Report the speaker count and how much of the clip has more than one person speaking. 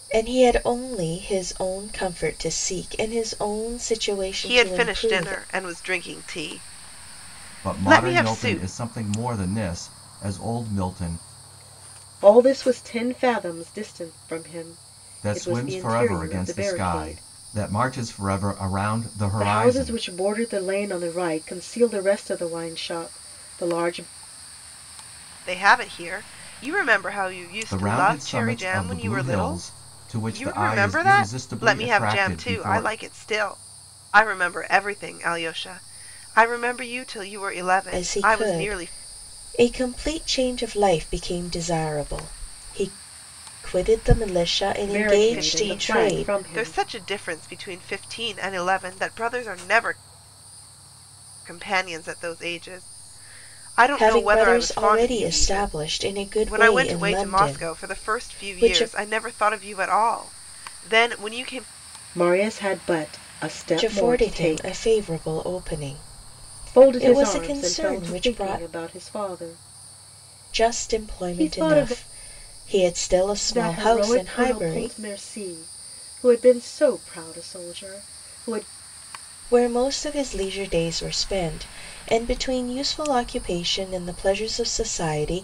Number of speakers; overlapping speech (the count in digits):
4, about 28%